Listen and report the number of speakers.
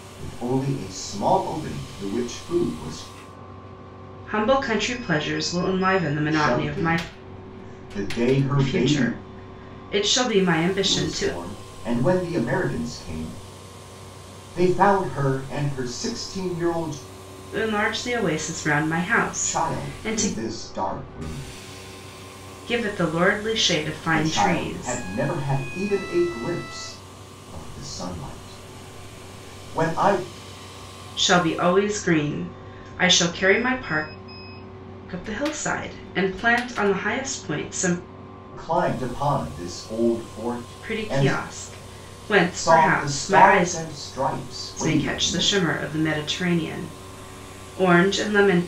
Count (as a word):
two